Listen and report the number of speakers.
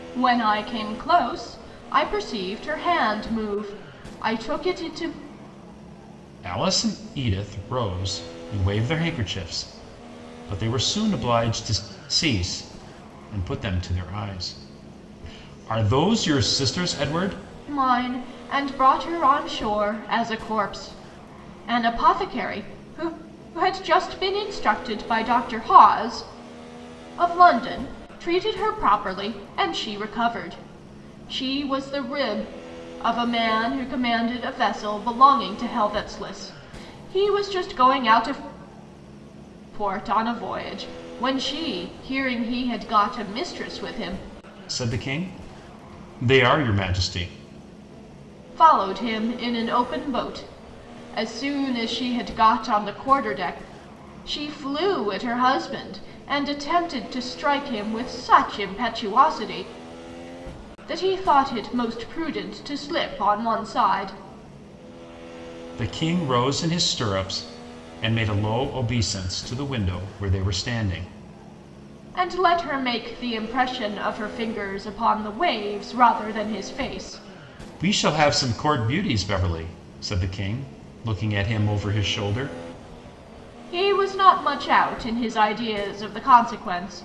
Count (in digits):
2